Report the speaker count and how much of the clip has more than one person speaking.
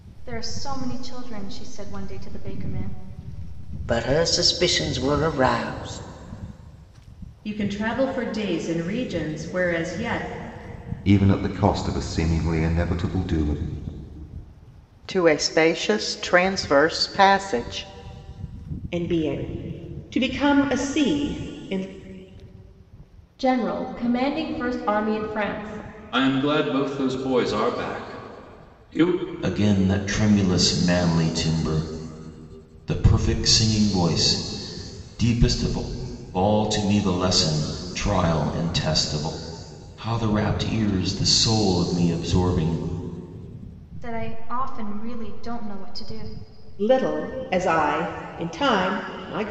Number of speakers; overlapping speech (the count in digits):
9, no overlap